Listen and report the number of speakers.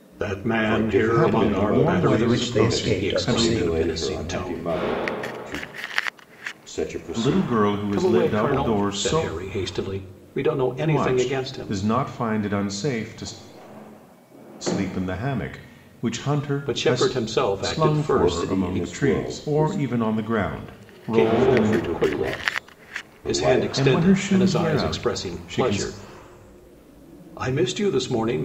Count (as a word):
four